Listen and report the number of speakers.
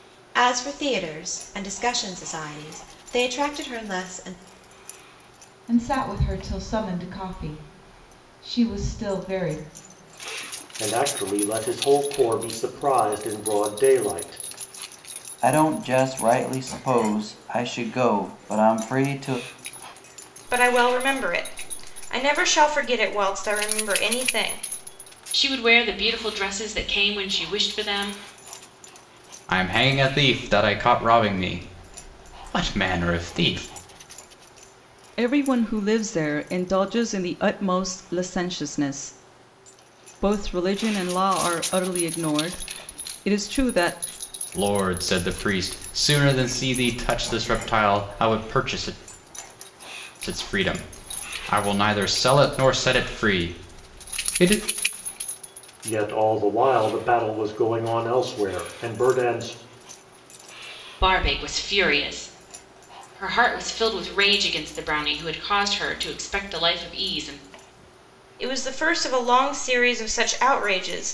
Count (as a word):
eight